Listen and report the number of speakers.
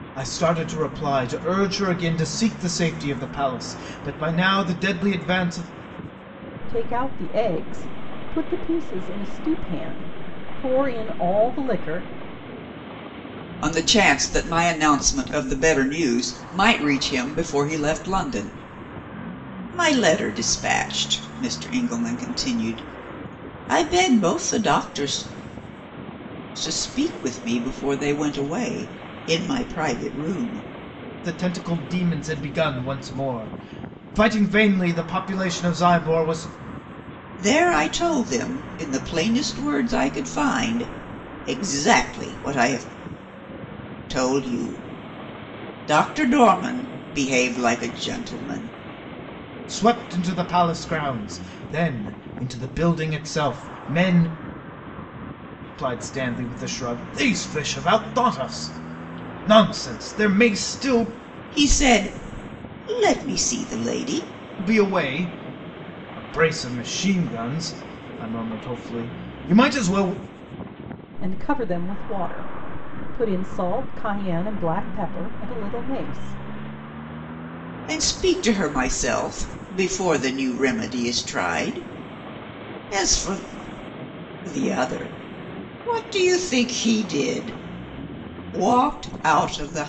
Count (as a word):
three